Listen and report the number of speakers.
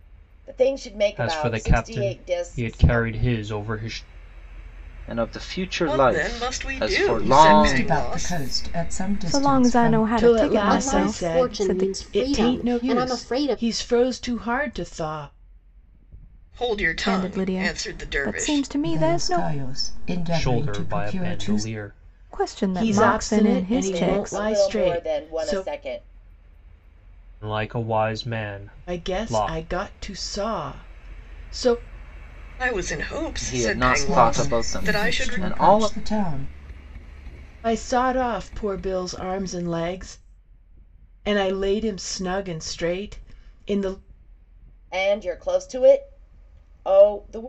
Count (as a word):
eight